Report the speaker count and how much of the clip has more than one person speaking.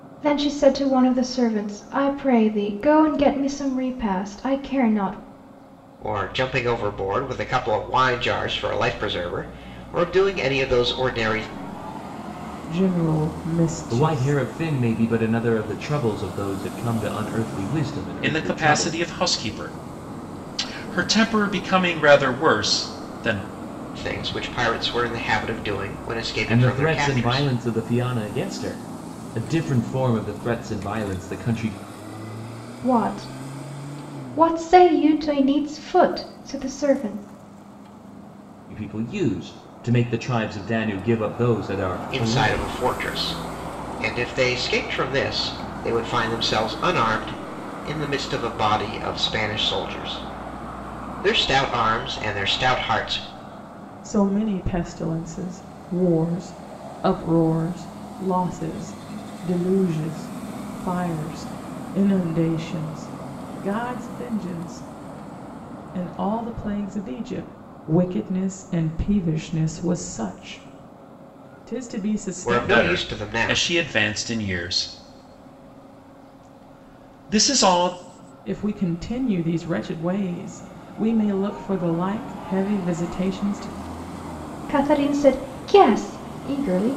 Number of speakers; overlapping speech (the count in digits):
5, about 5%